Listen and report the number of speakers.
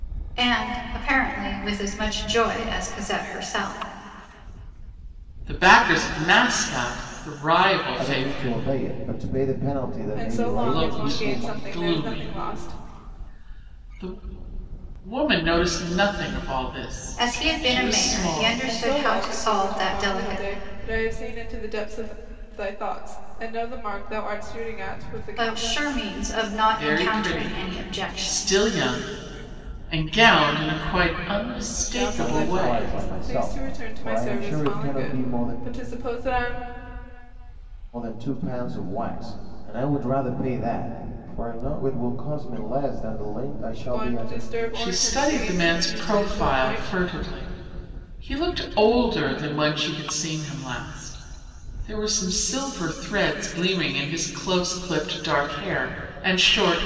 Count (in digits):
4